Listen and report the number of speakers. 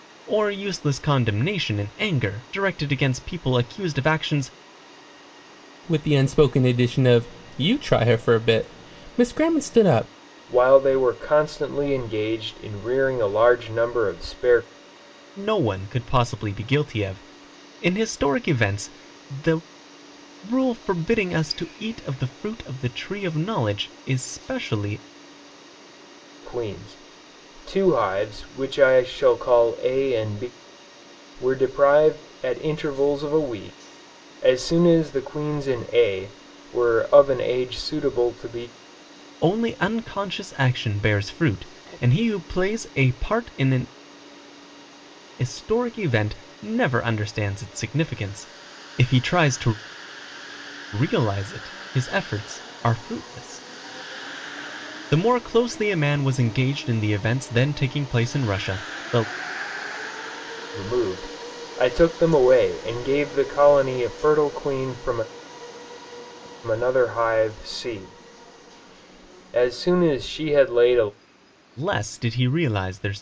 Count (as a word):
three